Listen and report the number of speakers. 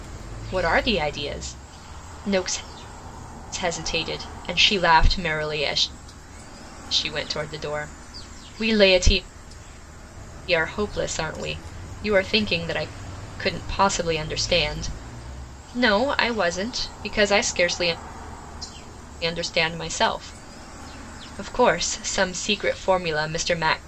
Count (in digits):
1